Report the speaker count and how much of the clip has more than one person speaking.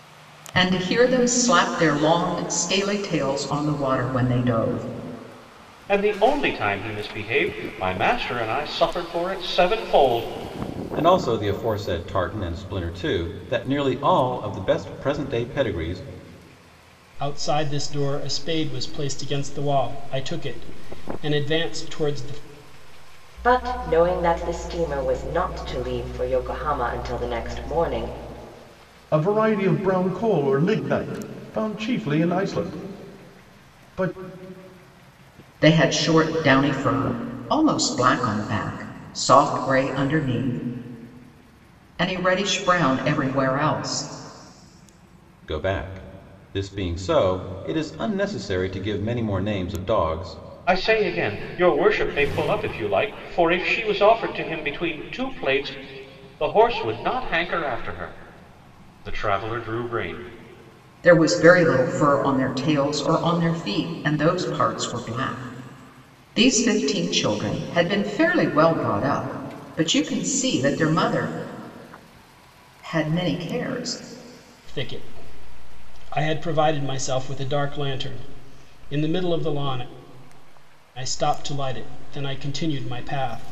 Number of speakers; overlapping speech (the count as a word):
six, no overlap